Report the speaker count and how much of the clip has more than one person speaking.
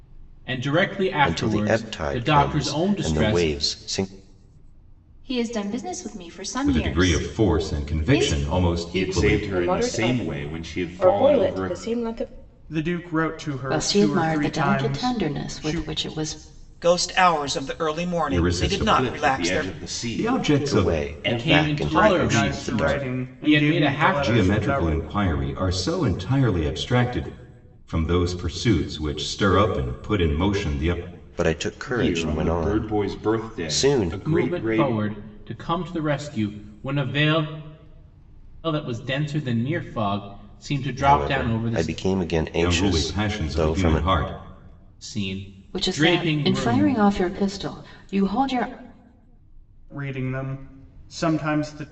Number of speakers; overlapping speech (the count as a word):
nine, about 43%